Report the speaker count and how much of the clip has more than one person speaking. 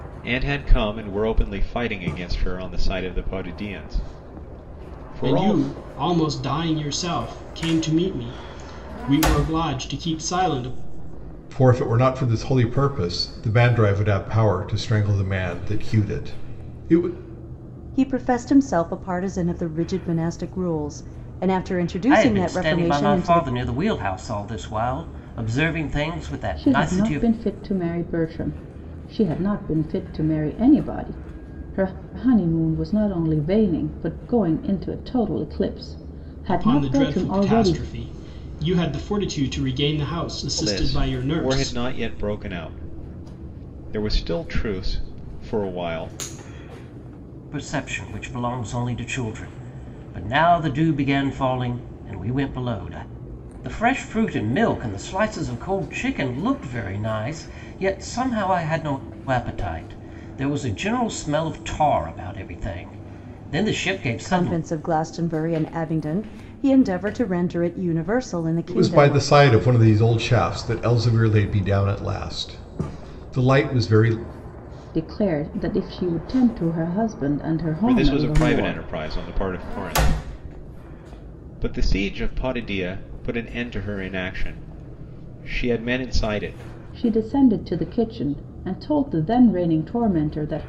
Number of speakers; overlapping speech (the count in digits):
6, about 8%